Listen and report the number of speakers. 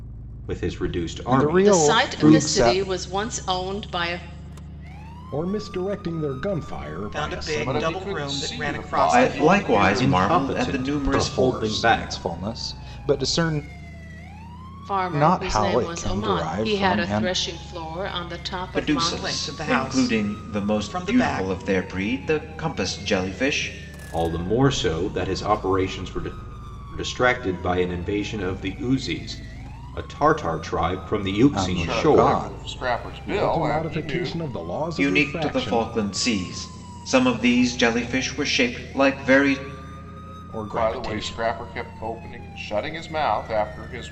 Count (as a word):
seven